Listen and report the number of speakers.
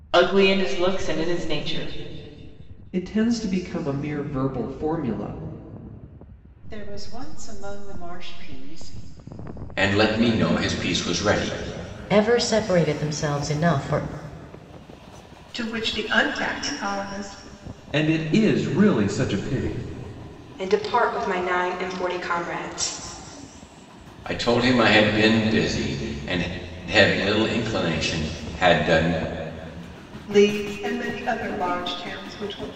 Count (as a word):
eight